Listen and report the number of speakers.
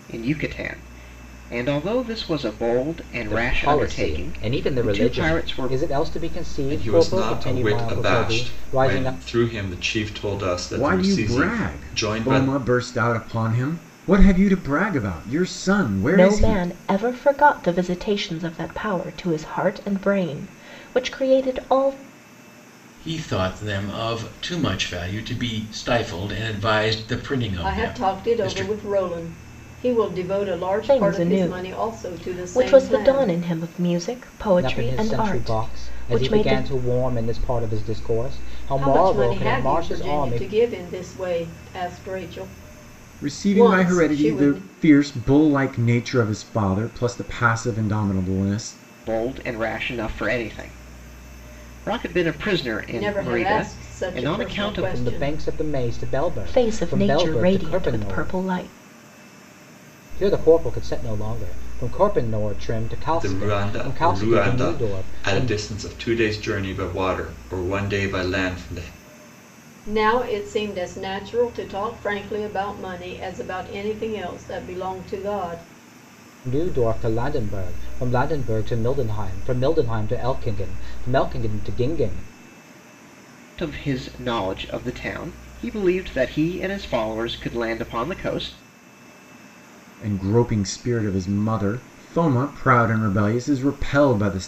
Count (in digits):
7